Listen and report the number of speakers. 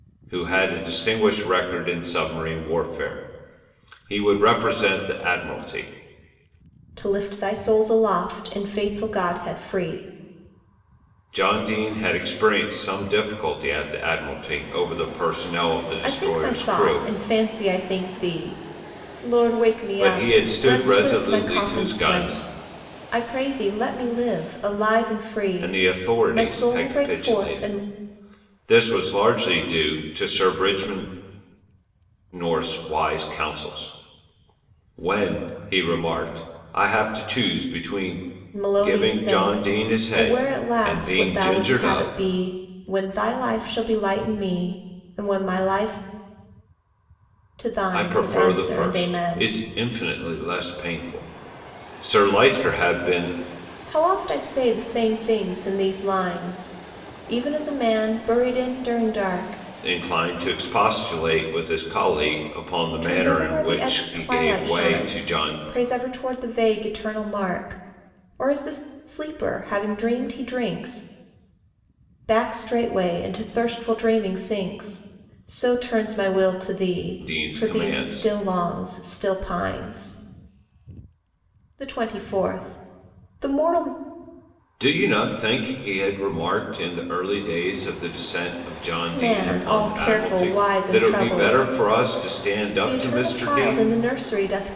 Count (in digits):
2